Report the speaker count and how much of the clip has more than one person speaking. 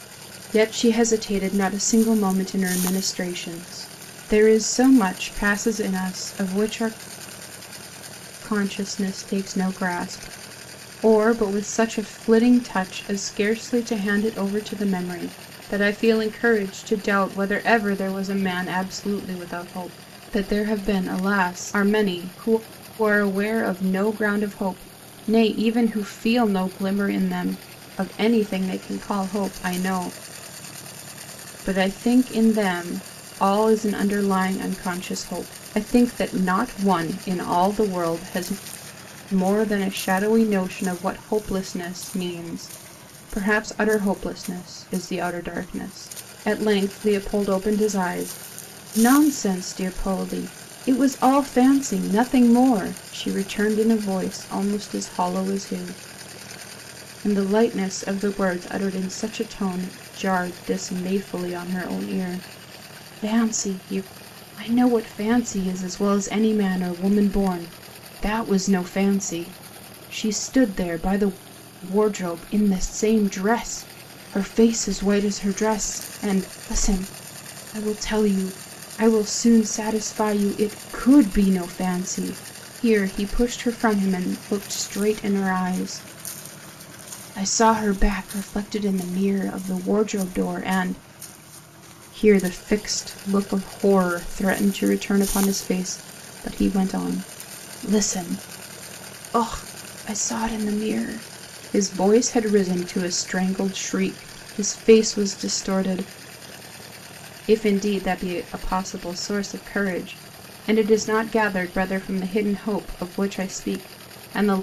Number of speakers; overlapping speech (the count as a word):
one, no overlap